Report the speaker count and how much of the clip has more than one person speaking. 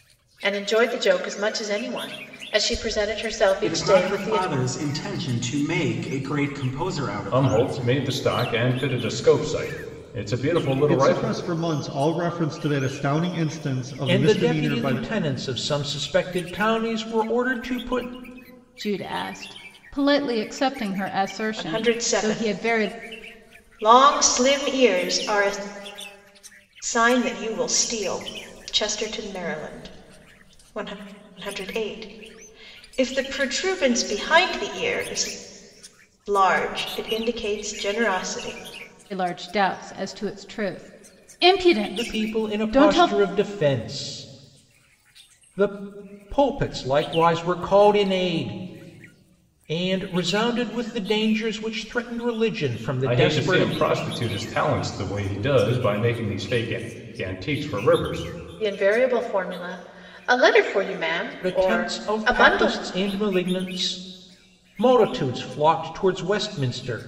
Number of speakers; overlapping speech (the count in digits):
7, about 11%